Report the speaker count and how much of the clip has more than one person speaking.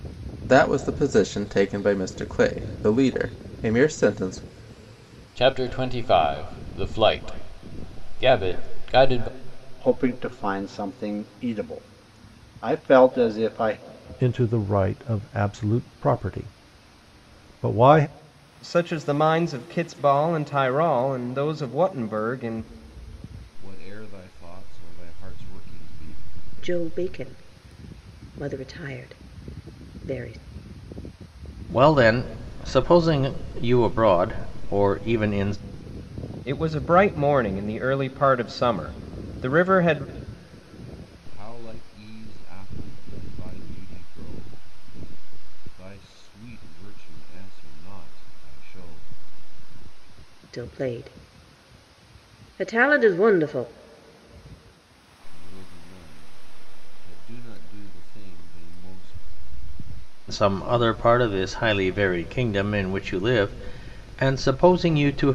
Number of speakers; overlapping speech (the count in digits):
8, no overlap